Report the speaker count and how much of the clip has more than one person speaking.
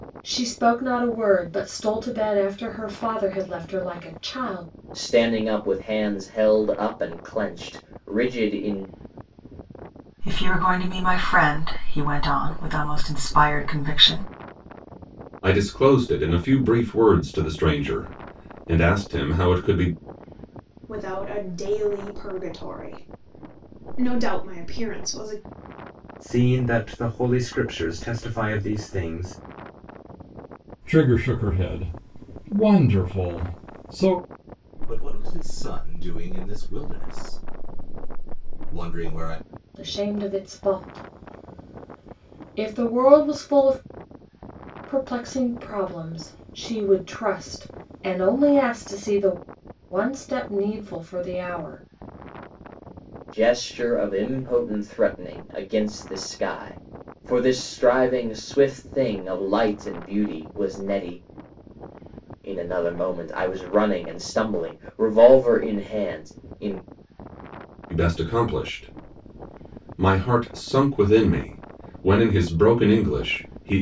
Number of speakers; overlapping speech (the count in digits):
8, no overlap